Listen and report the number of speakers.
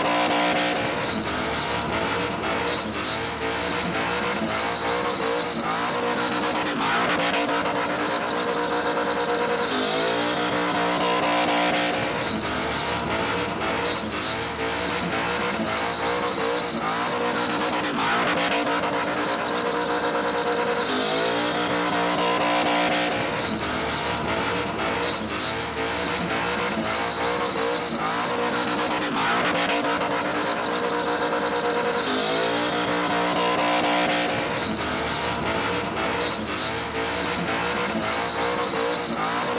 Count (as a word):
zero